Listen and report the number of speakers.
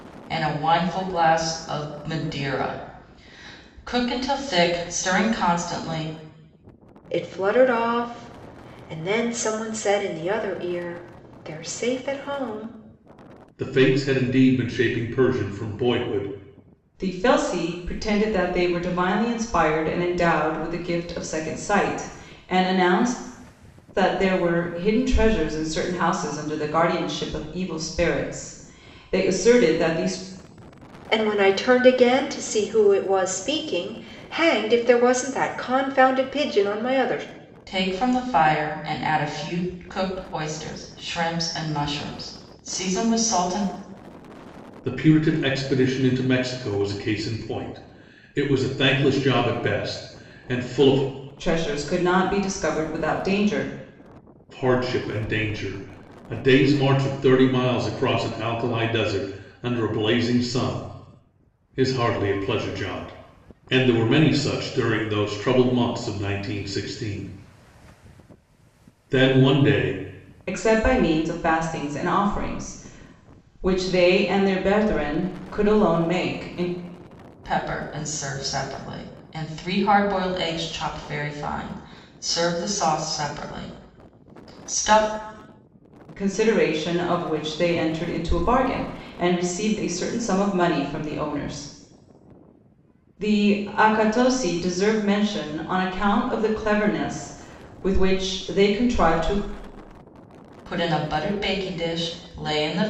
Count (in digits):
4